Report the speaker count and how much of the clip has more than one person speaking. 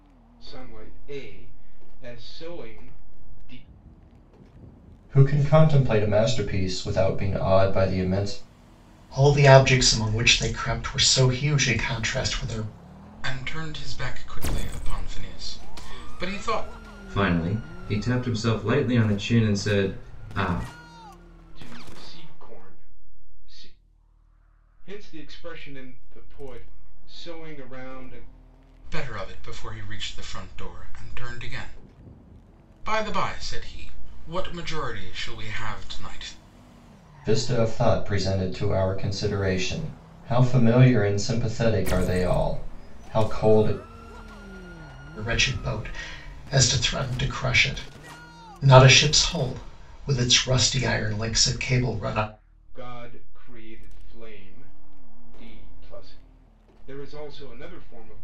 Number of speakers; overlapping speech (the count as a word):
five, no overlap